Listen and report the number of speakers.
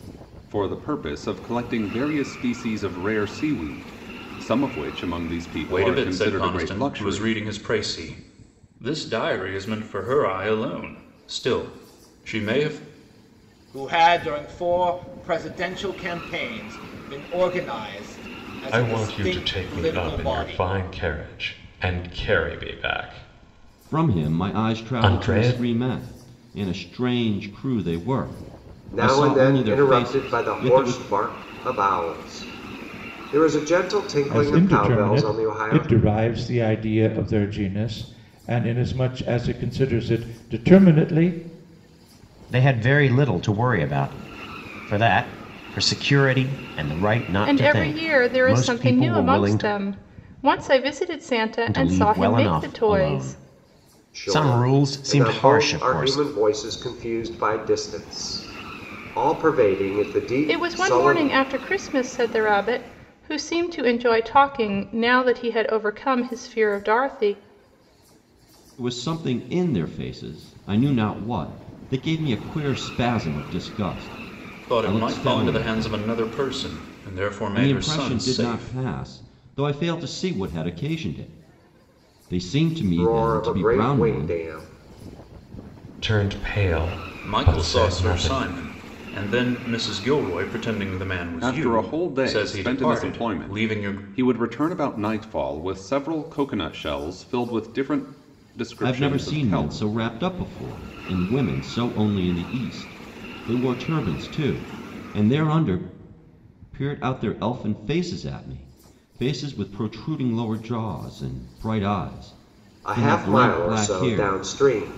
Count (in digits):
9